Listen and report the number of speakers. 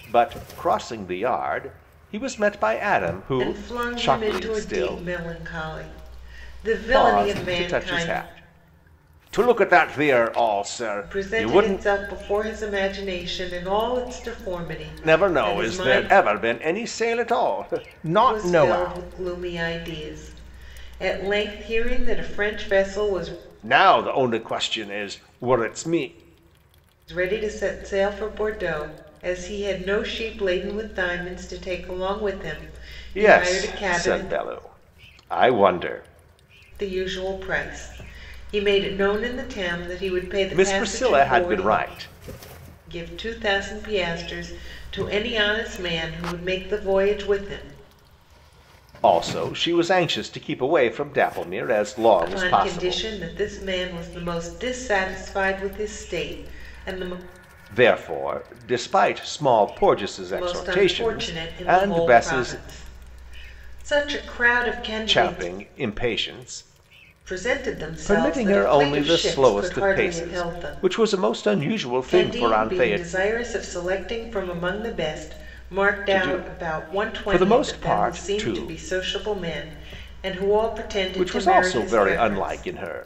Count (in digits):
2